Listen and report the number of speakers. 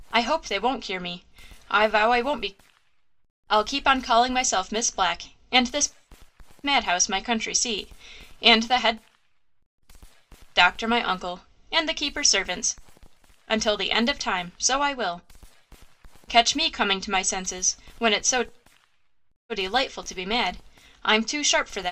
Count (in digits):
1